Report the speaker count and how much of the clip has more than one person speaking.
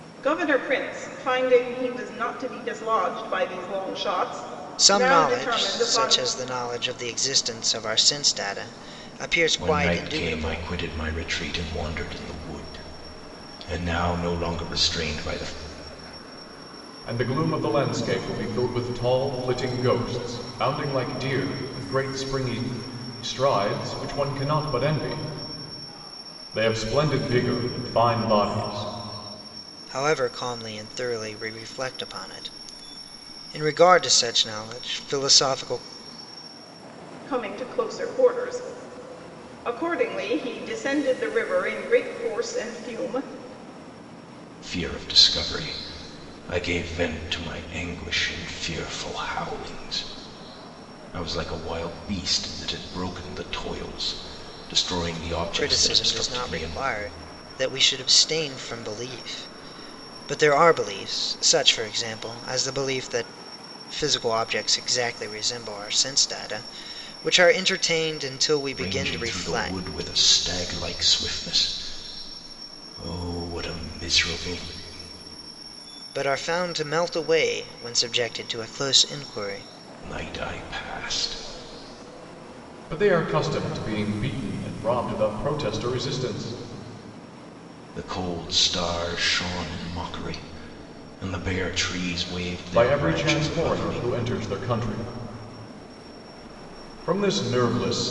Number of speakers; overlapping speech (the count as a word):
four, about 7%